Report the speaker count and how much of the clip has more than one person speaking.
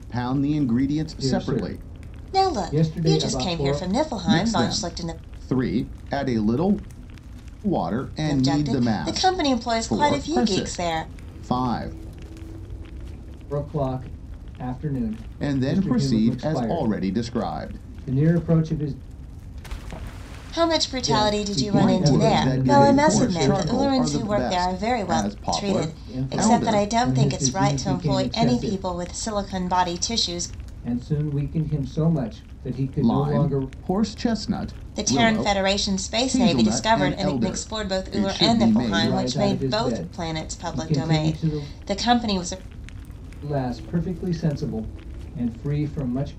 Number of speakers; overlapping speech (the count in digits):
3, about 49%